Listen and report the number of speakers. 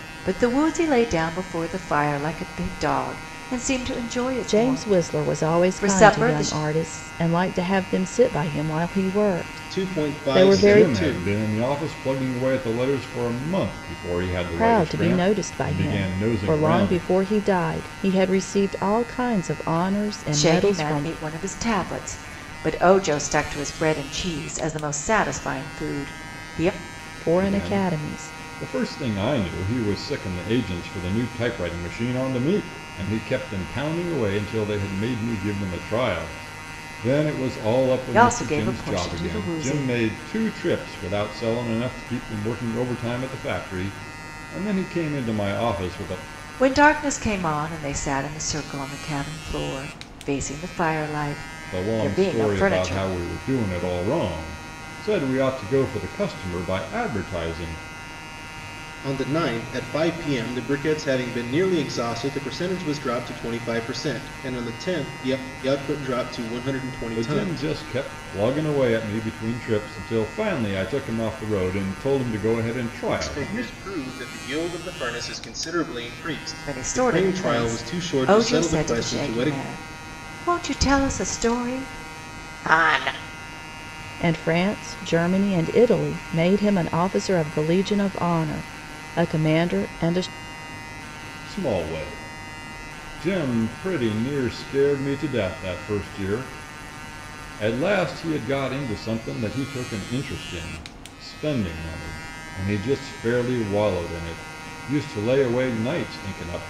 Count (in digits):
4